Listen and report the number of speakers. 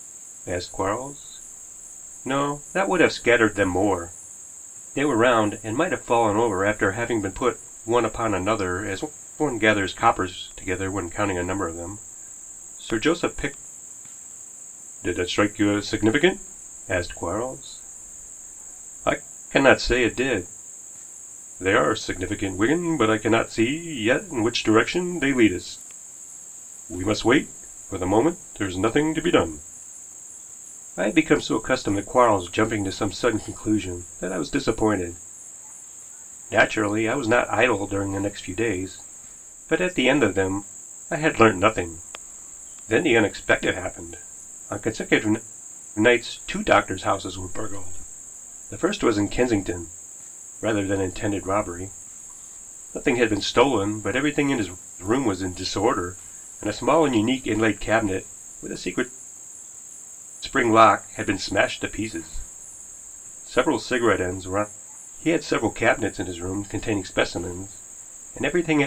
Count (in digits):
1